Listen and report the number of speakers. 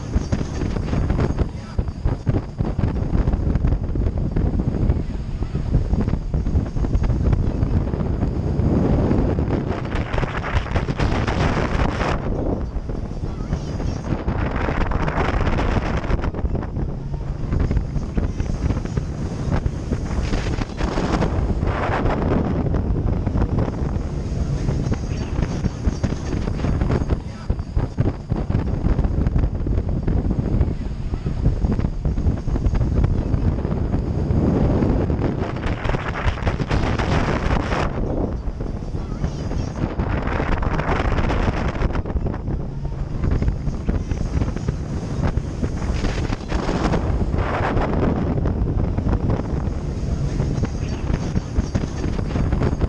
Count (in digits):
0